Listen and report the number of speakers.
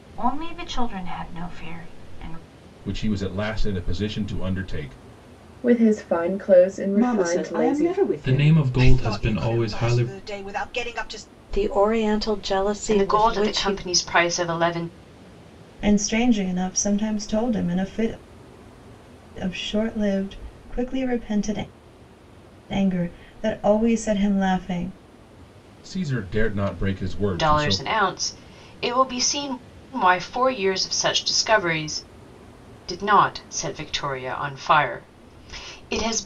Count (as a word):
nine